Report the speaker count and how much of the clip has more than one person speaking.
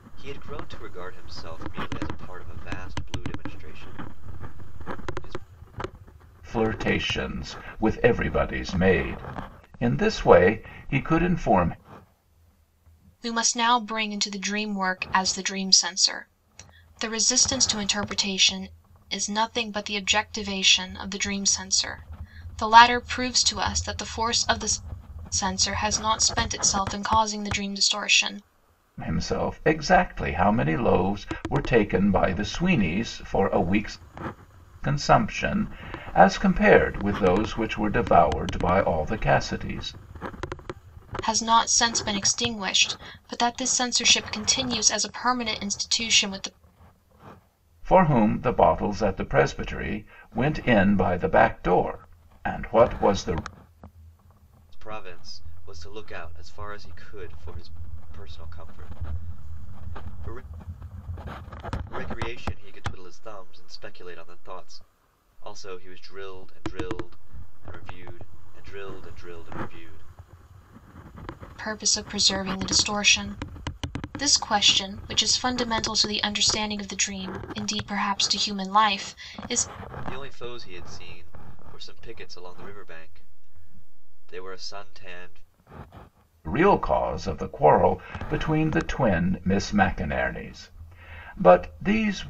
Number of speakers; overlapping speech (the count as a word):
three, no overlap